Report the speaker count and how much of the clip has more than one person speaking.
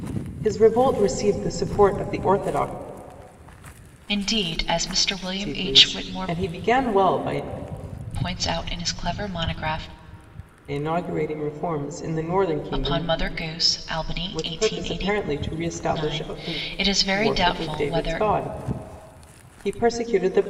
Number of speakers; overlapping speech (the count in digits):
2, about 20%